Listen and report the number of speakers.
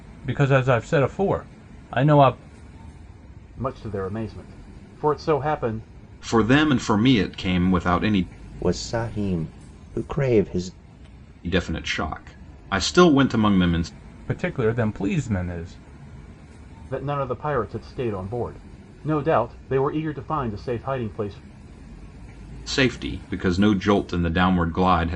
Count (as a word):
four